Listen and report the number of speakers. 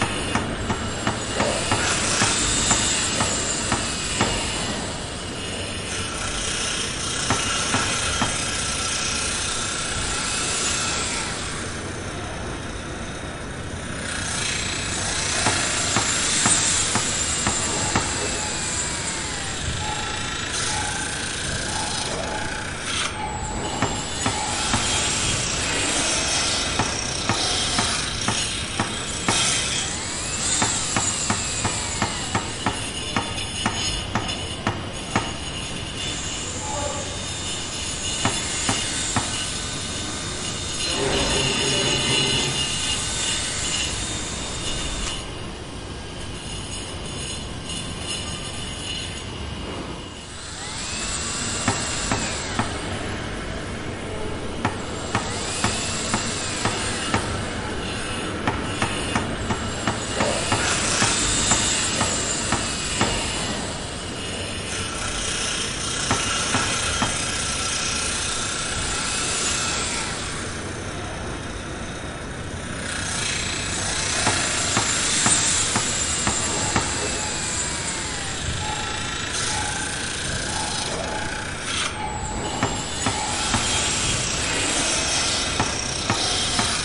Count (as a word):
zero